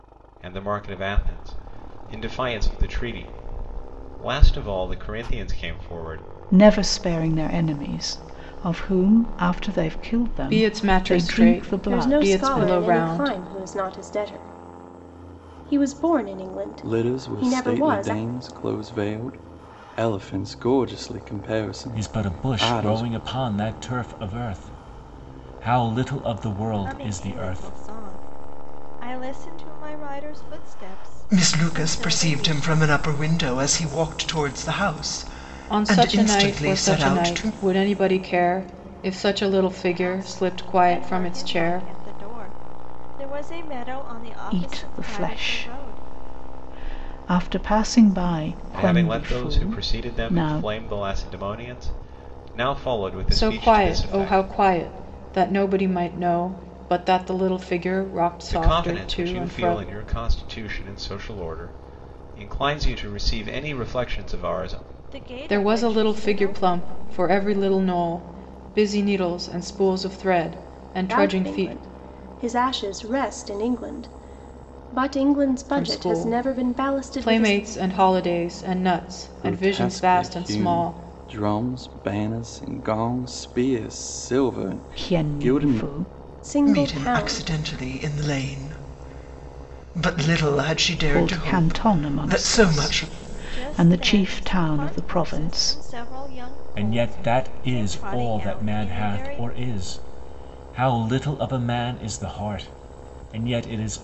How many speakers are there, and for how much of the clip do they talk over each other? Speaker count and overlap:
8, about 32%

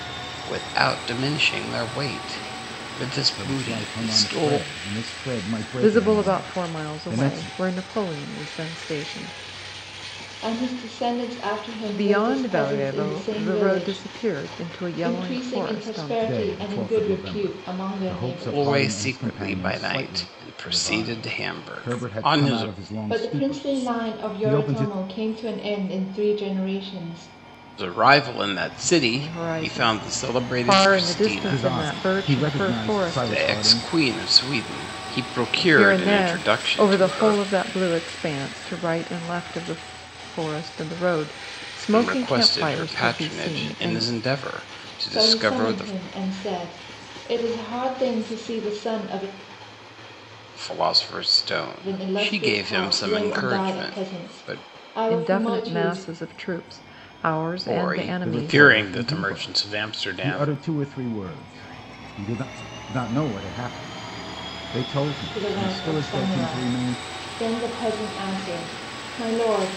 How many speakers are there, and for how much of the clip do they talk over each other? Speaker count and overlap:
4, about 47%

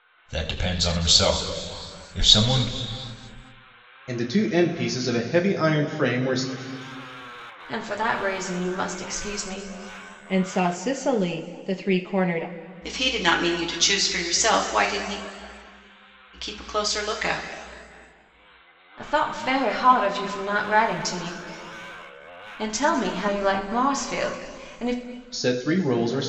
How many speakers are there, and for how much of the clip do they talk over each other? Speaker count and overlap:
5, no overlap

